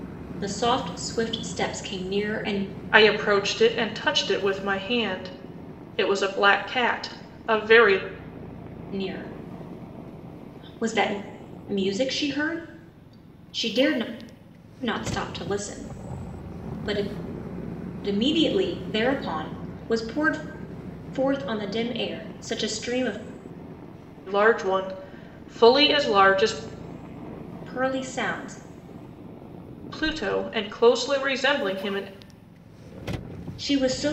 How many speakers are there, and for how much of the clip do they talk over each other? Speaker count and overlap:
2, no overlap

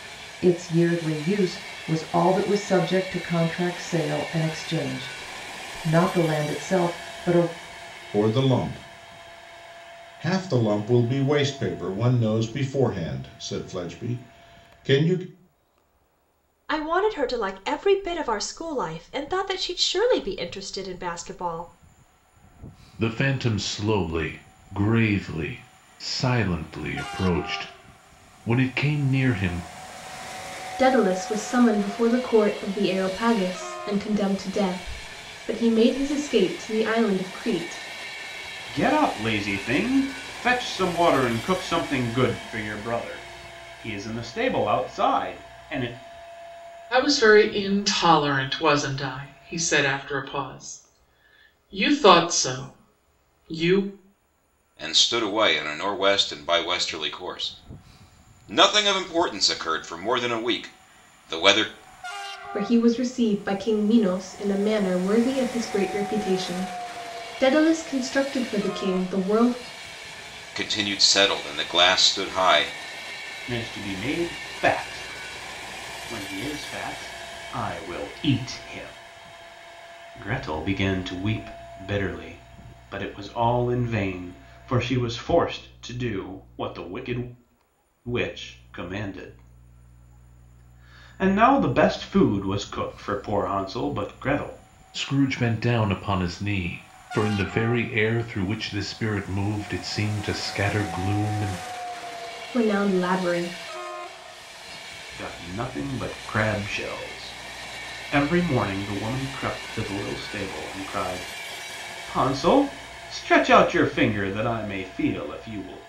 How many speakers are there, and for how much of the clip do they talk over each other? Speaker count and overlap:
8, no overlap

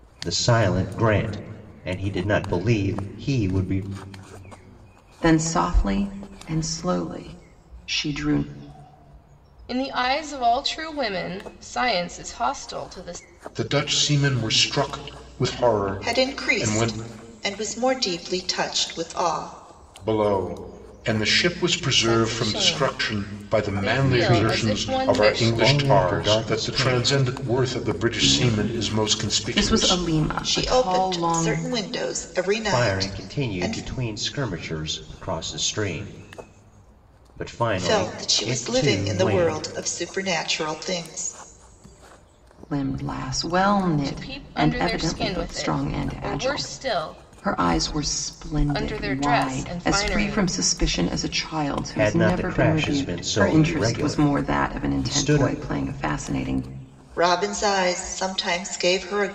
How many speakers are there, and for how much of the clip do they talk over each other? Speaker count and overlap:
5, about 36%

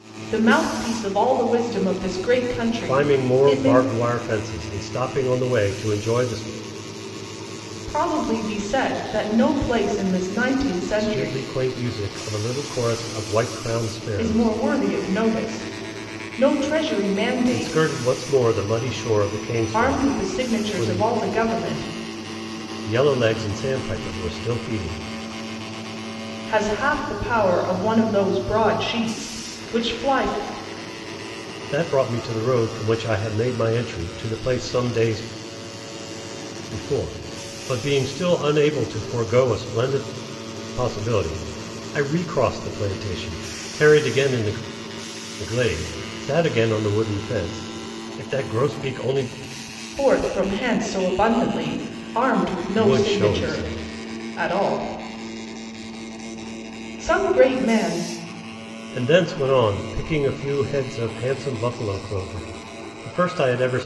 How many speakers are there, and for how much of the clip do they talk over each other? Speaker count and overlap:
2, about 7%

